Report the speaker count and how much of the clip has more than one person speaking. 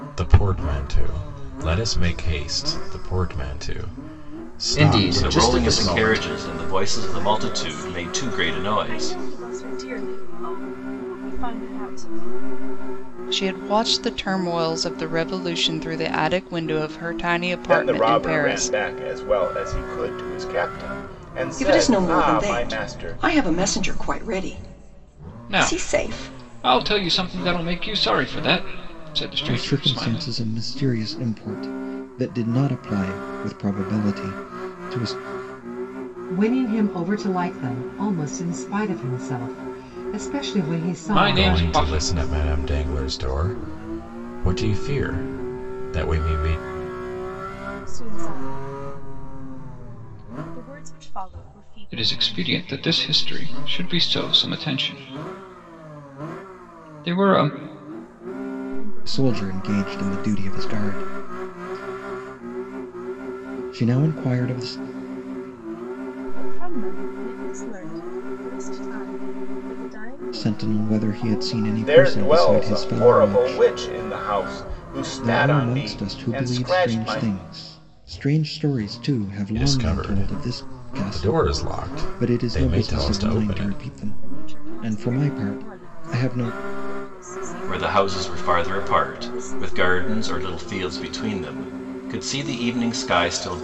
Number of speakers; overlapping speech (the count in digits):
10, about 28%